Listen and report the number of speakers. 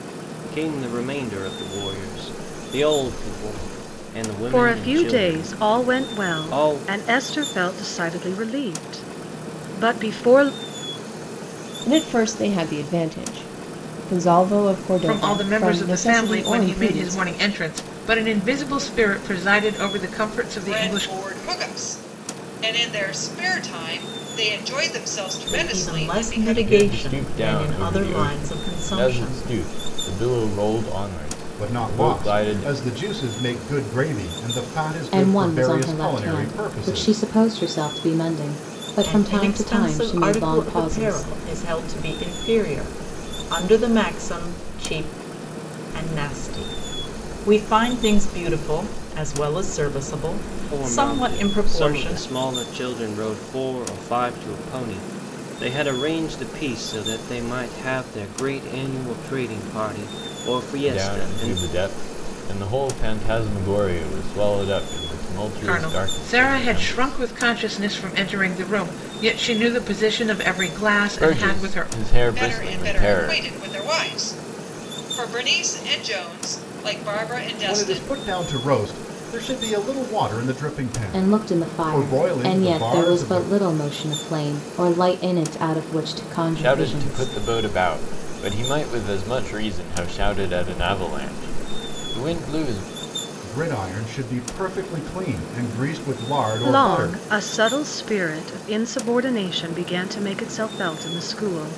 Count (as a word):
nine